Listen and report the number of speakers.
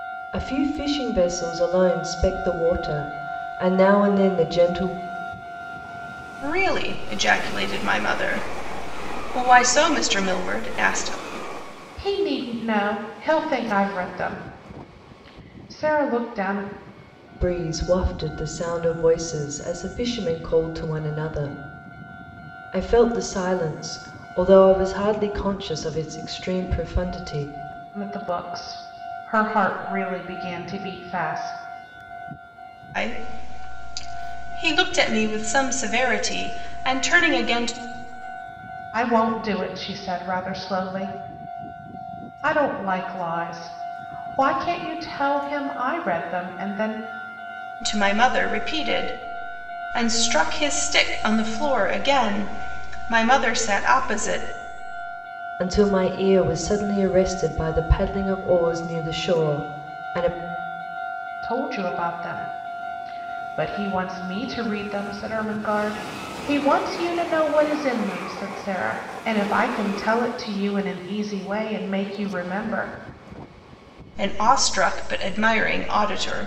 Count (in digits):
3